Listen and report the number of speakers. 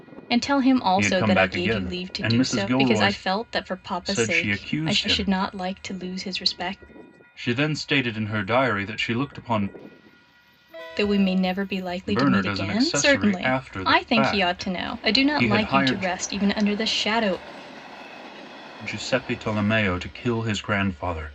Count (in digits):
2